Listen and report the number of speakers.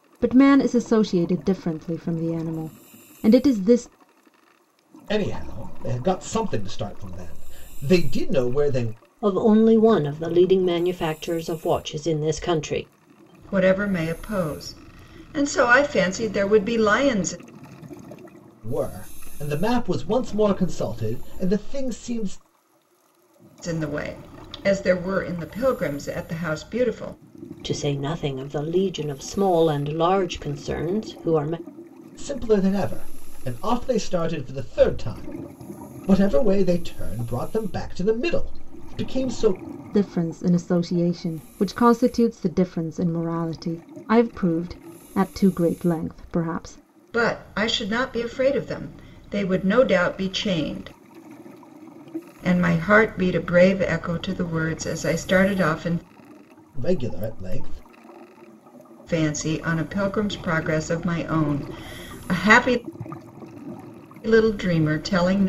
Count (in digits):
4